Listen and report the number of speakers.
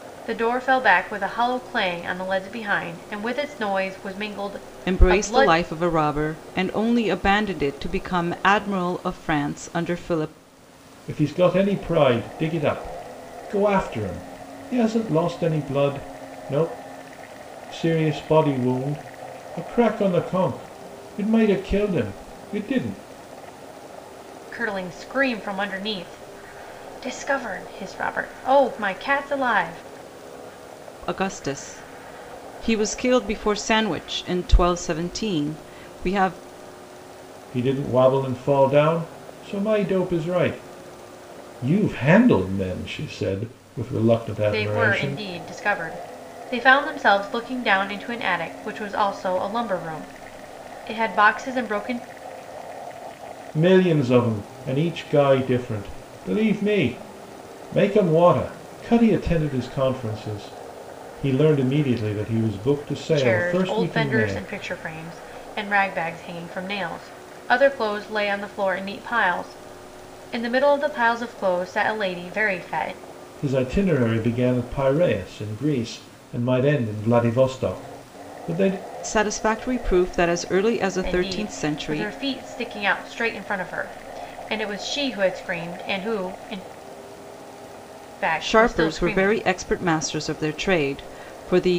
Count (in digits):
3